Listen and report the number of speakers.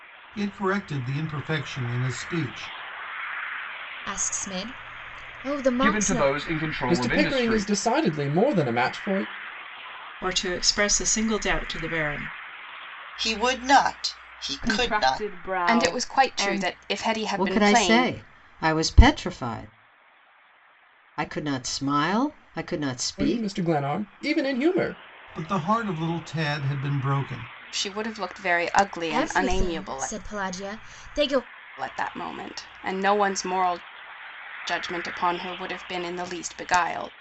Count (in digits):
9